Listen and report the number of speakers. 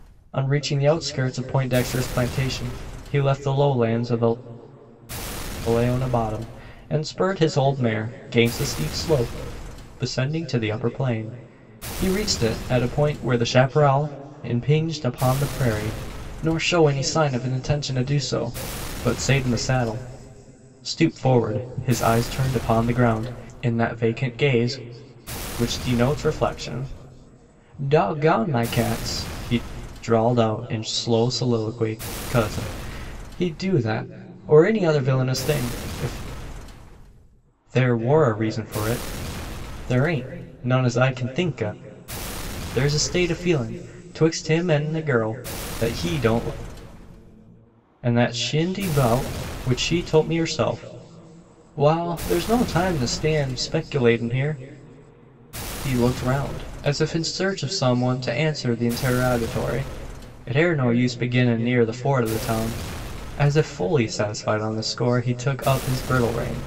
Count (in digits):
1